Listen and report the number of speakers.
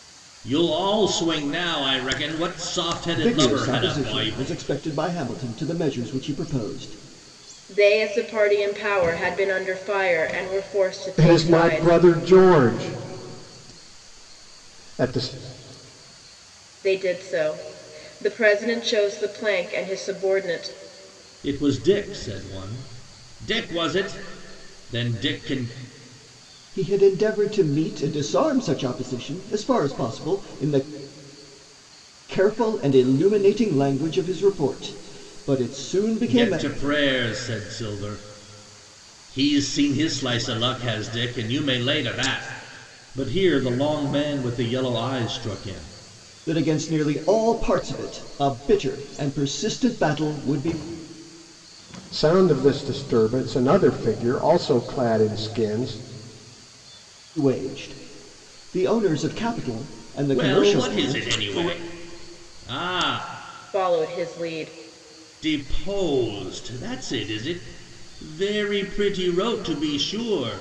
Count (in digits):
4